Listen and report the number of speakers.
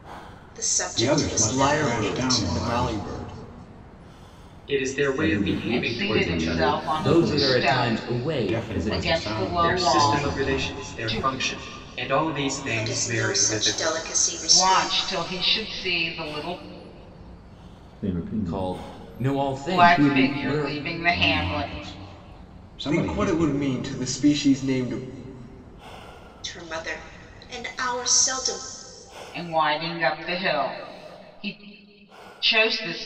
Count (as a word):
seven